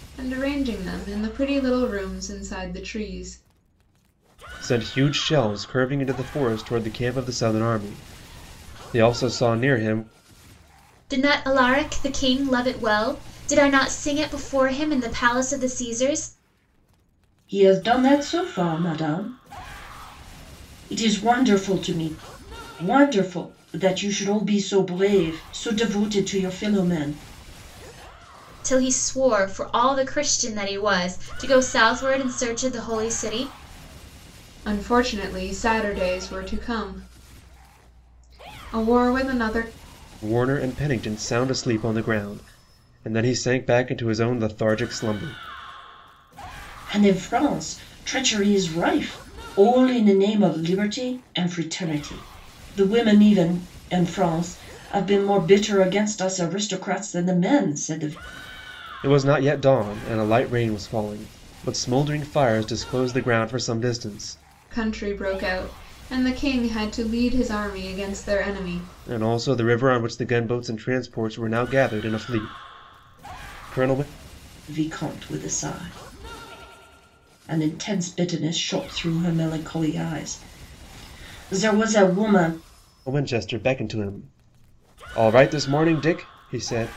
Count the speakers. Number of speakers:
4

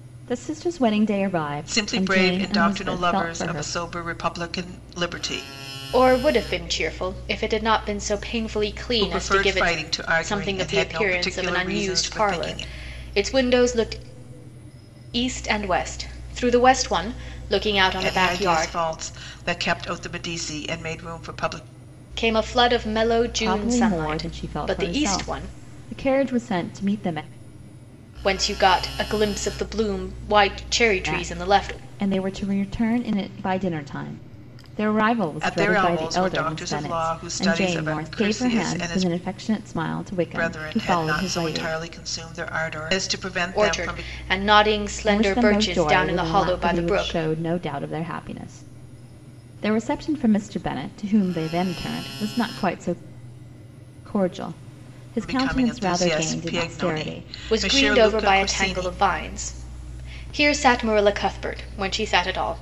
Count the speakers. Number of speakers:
3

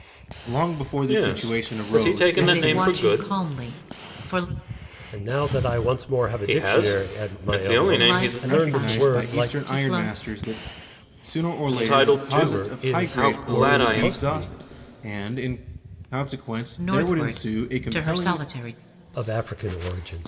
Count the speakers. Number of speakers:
4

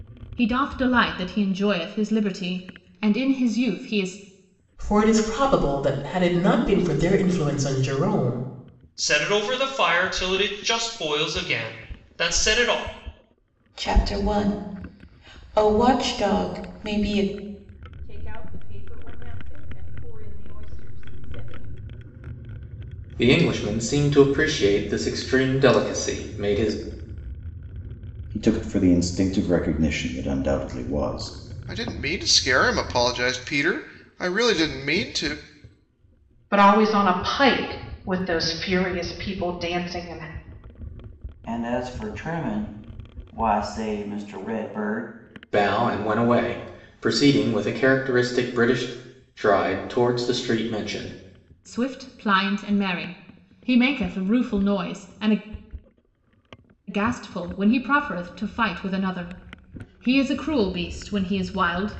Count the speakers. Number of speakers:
10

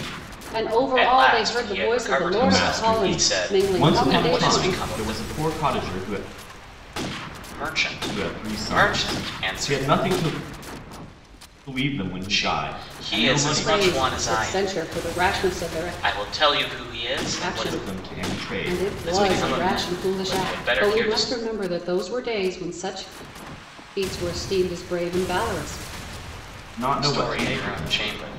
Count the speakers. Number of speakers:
3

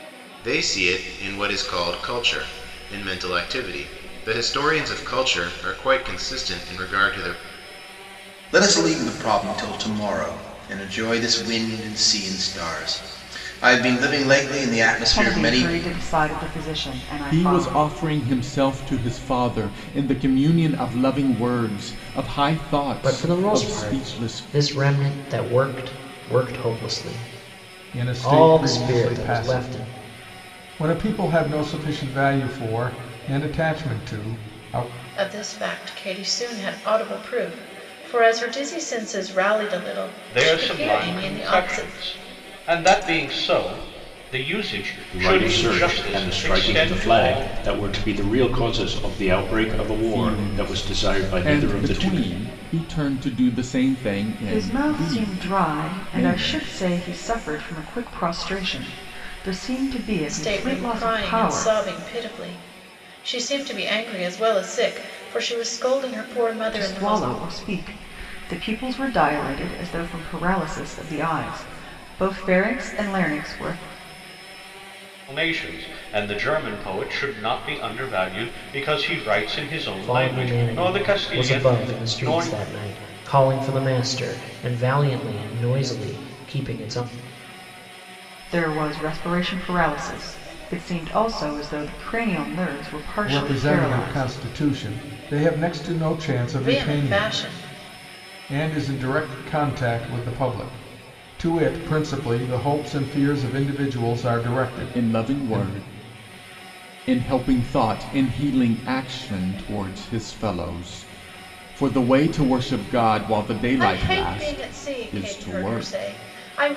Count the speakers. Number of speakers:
9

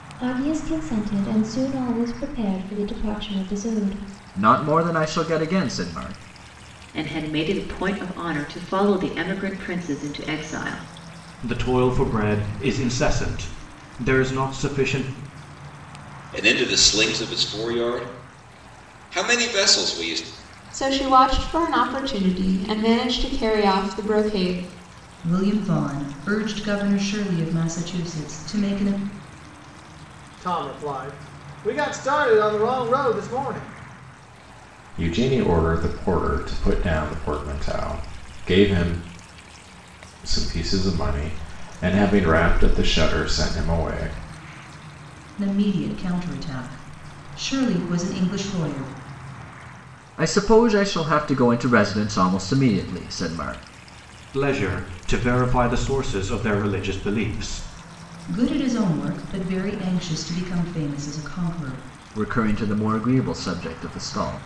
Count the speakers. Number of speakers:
9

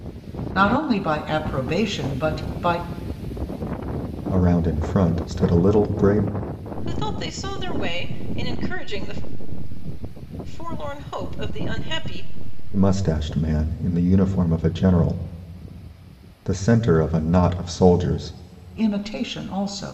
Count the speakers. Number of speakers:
3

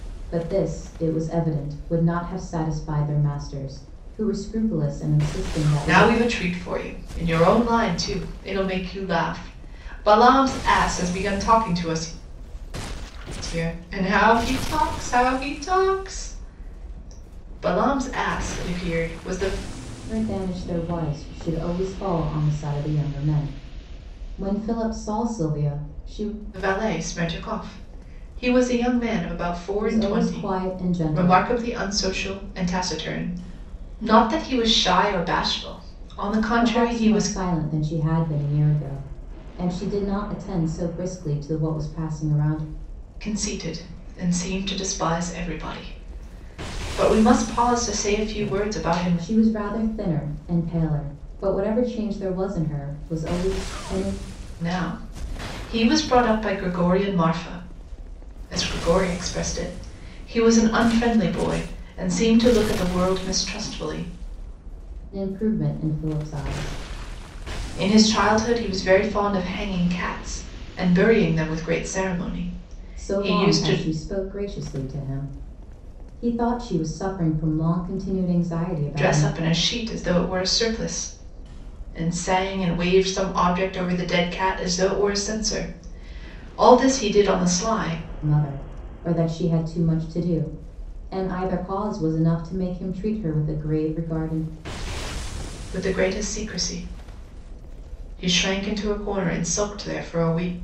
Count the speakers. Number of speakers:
2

